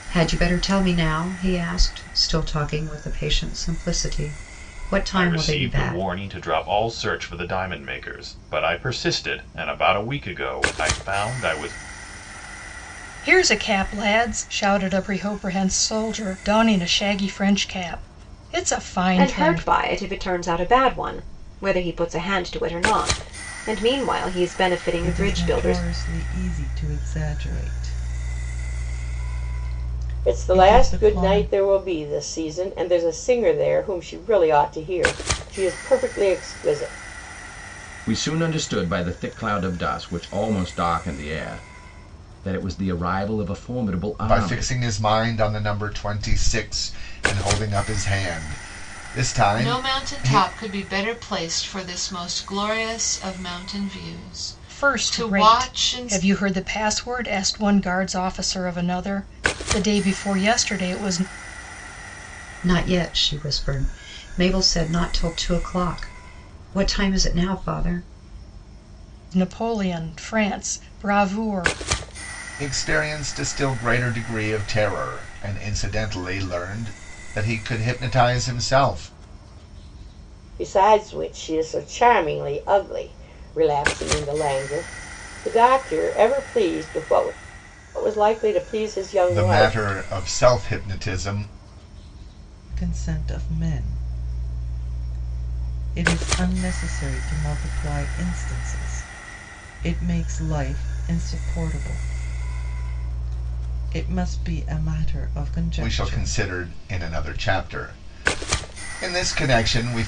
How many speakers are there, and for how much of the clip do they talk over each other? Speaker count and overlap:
nine, about 7%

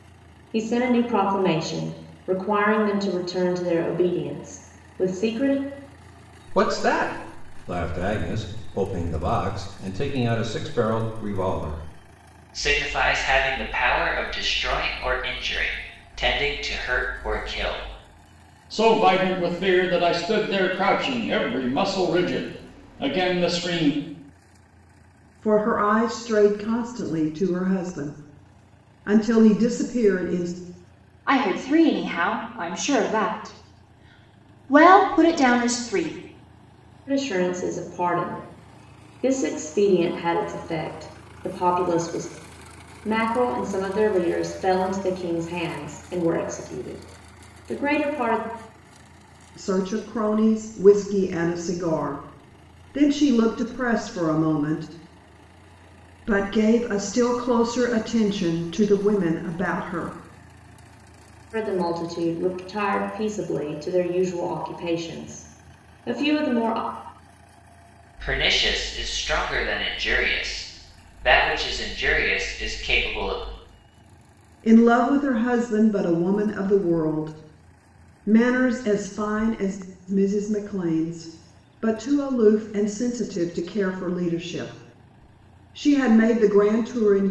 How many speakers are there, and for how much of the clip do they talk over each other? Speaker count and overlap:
six, no overlap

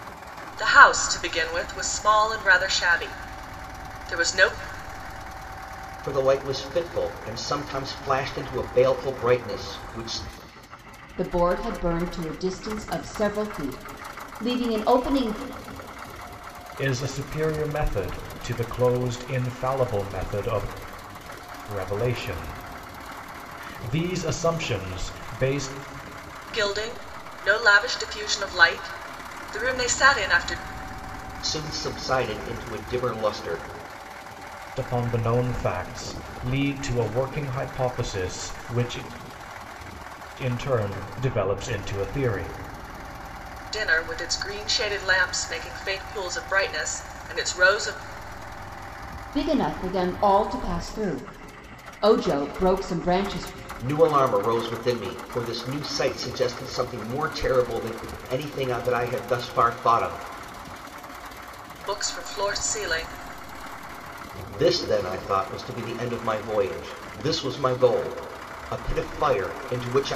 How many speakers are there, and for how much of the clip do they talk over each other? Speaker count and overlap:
four, no overlap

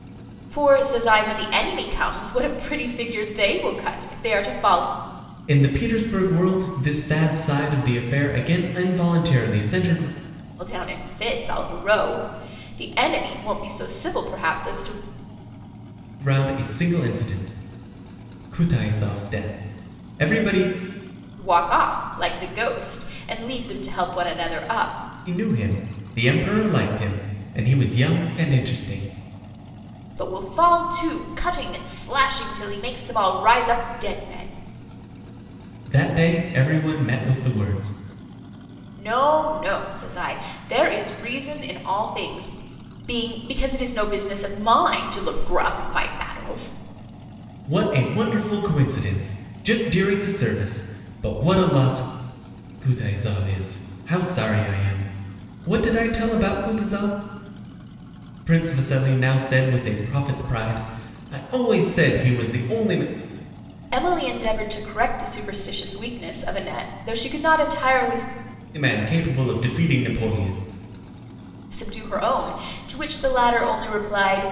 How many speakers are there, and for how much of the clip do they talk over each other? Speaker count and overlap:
two, no overlap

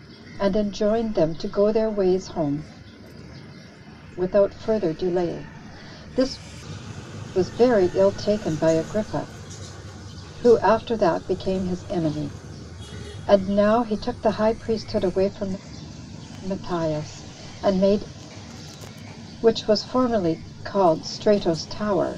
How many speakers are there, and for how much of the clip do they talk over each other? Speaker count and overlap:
one, no overlap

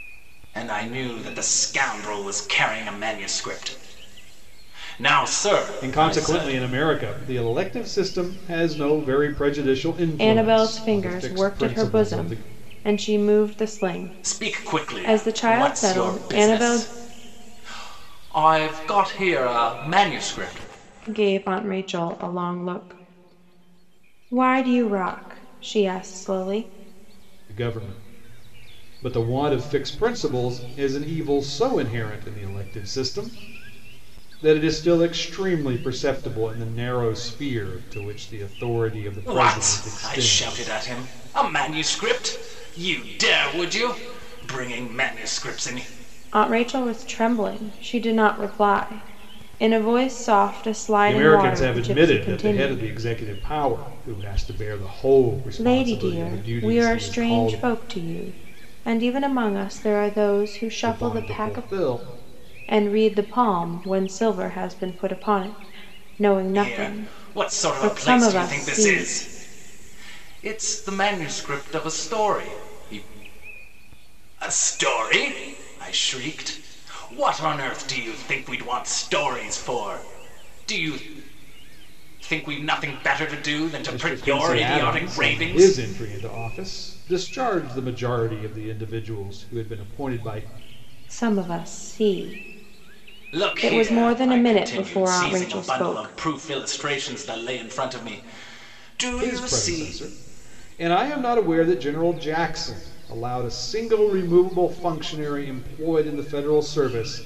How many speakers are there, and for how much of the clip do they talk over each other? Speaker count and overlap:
three, about 19%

